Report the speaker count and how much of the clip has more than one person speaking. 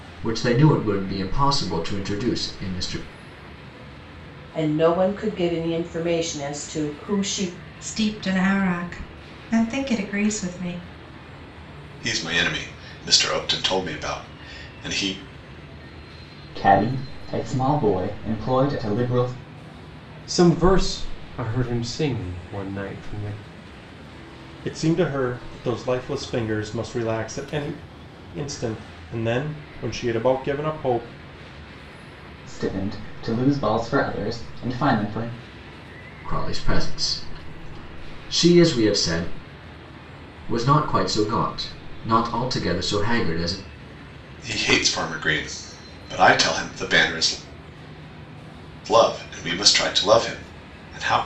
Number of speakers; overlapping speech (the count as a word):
seven, no overlap